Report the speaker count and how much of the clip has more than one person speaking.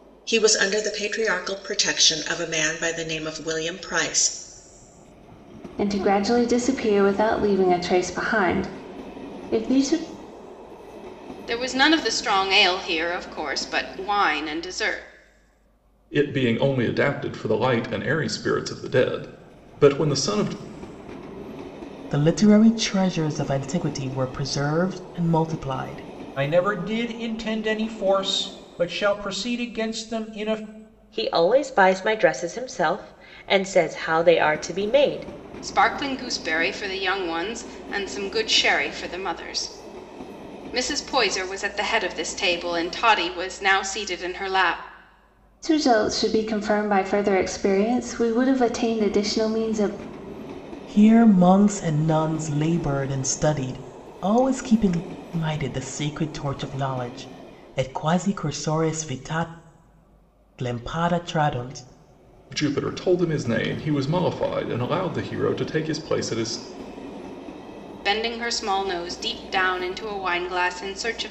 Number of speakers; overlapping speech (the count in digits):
7, no overlap